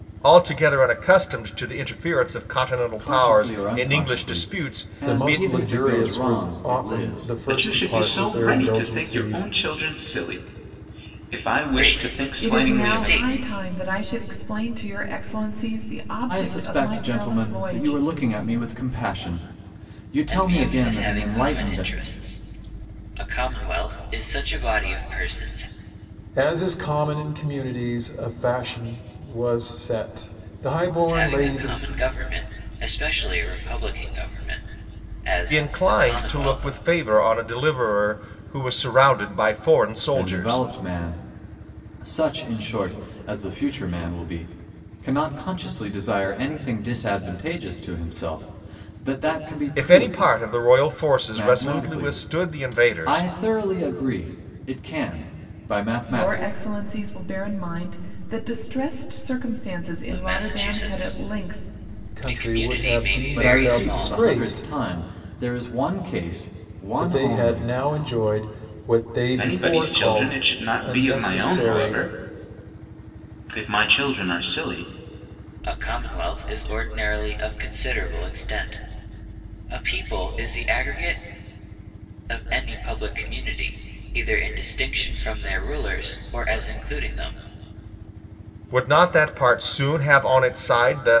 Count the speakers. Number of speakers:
6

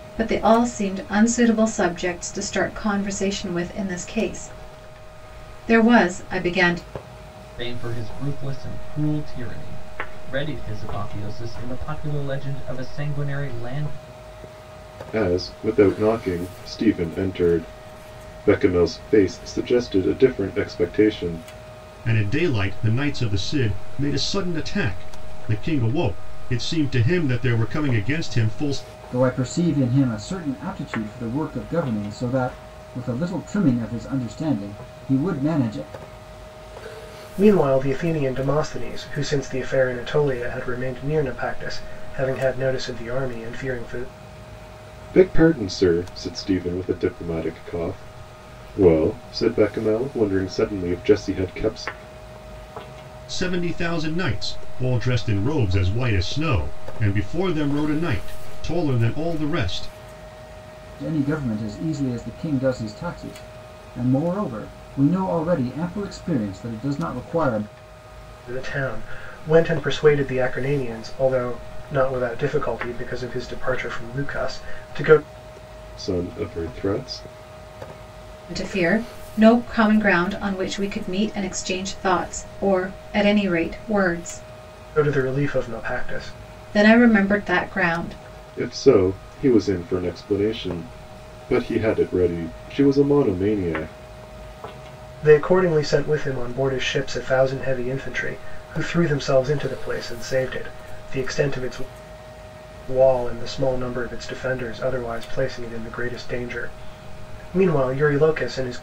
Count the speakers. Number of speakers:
6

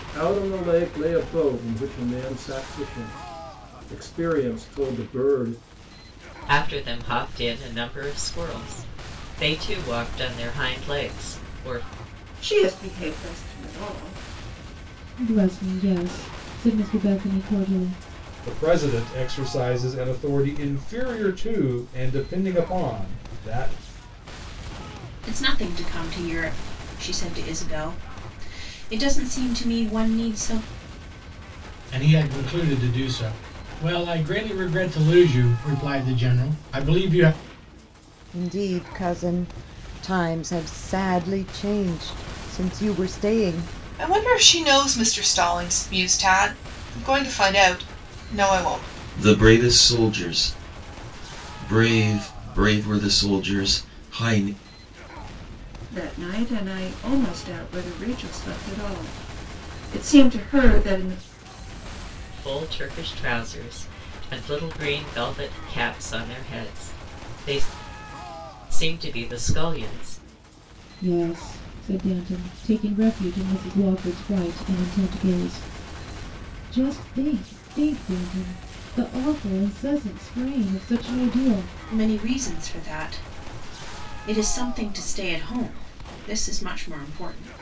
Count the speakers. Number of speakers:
10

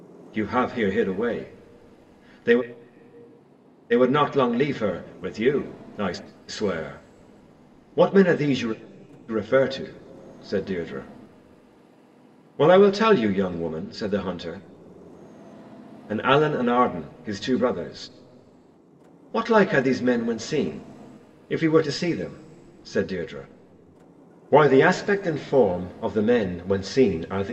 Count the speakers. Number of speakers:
1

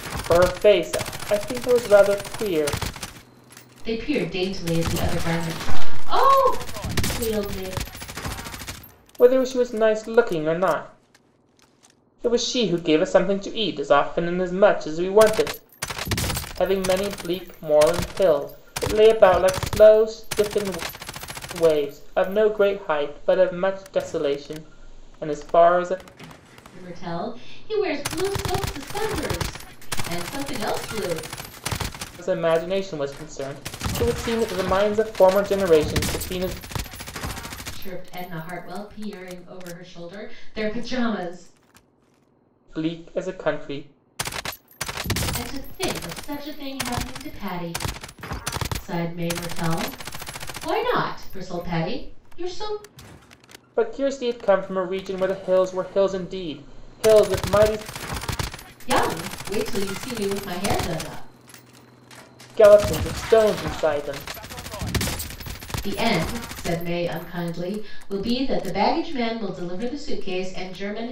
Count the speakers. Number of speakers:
2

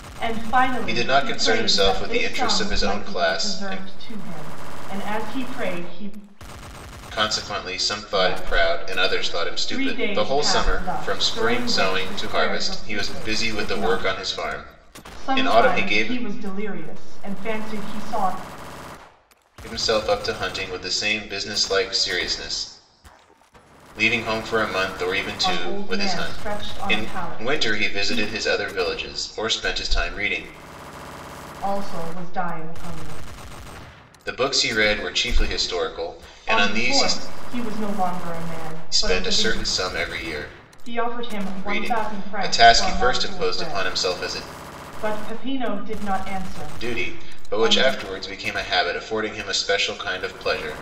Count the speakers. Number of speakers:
2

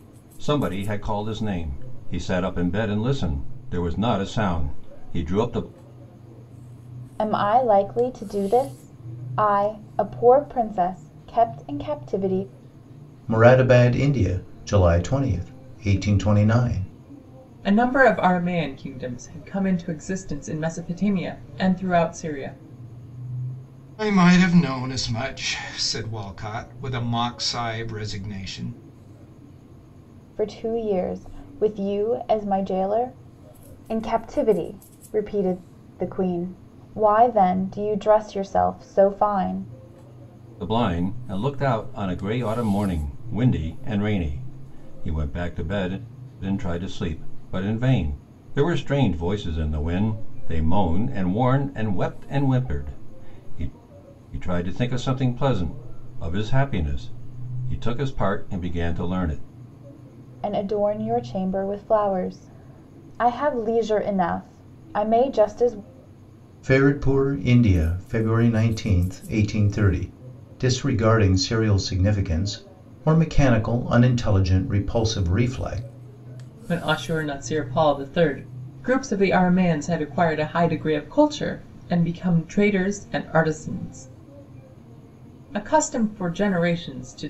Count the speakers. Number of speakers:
5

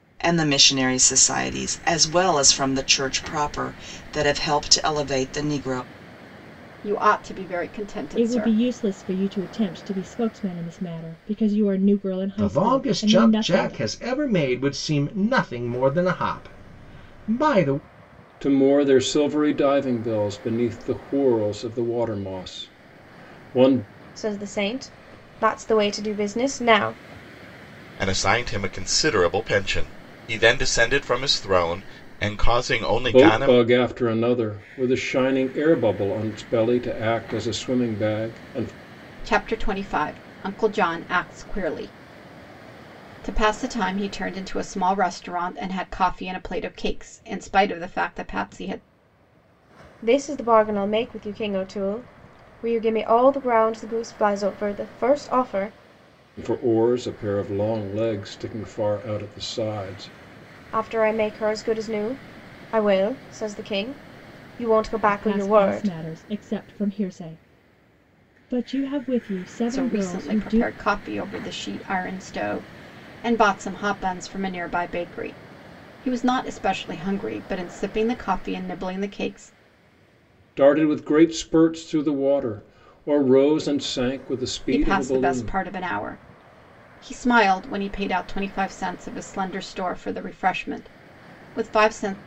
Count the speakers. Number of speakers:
7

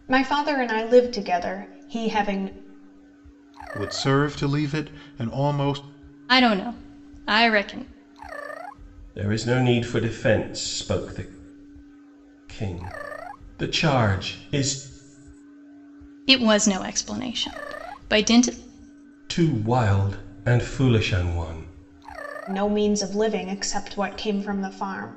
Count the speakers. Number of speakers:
4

